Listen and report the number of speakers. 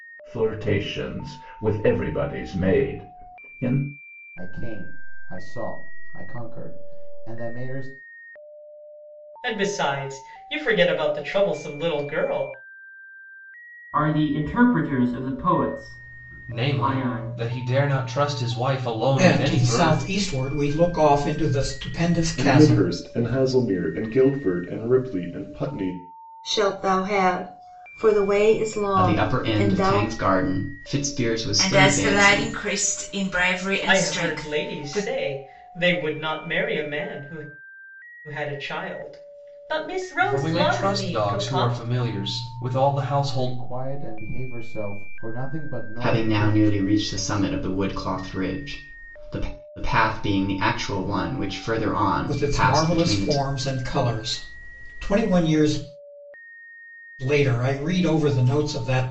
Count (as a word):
ten